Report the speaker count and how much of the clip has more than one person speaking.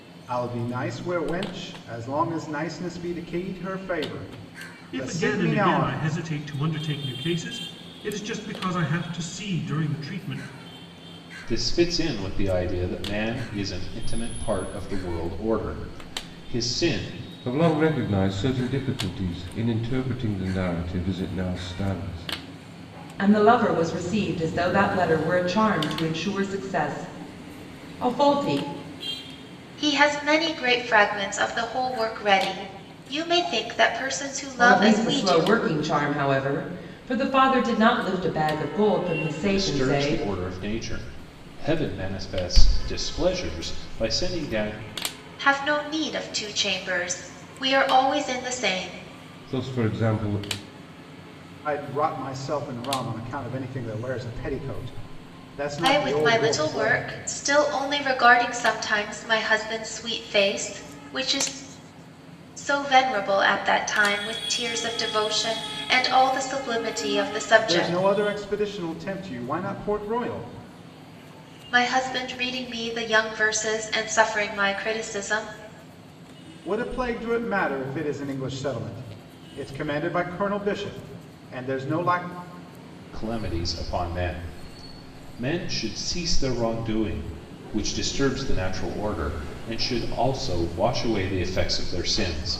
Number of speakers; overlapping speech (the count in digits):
6, about 5%